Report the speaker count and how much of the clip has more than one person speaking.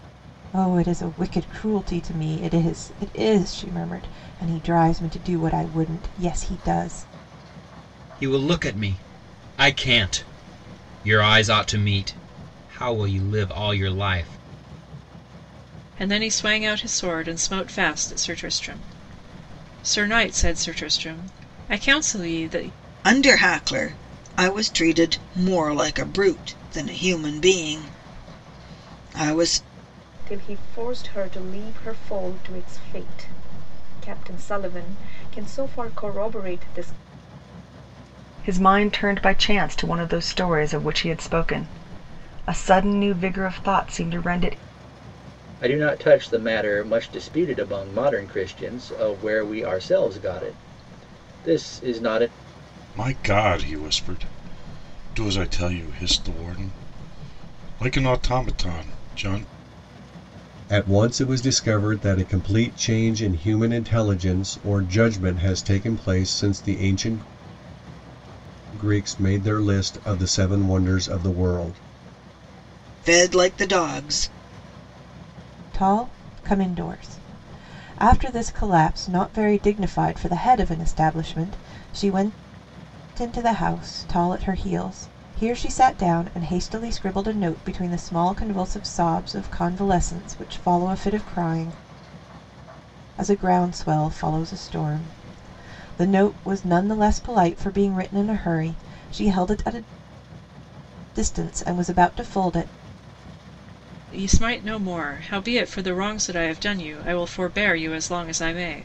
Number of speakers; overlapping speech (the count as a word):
nine, no overlap